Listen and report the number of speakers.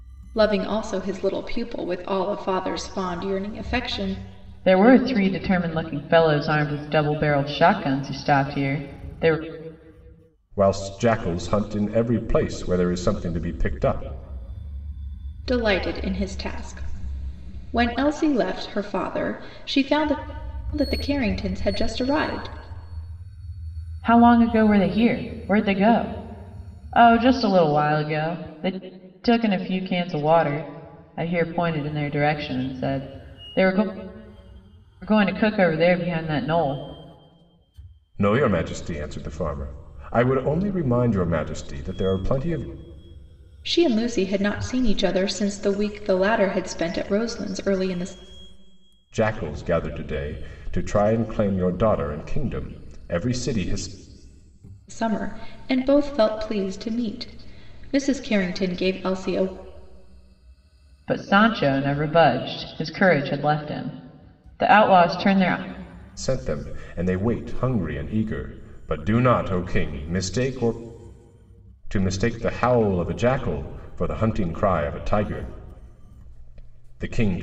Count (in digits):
3